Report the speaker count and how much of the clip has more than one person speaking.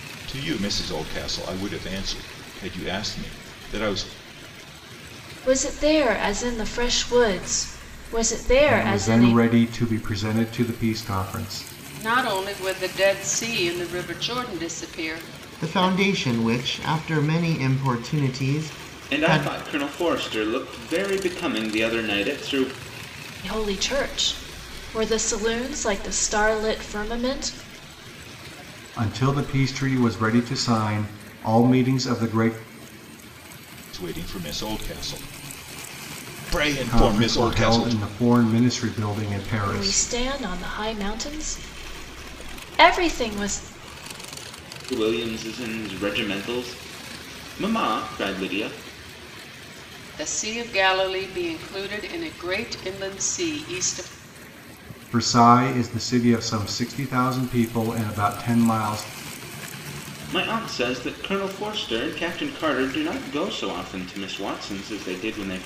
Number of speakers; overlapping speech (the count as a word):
six, about 5%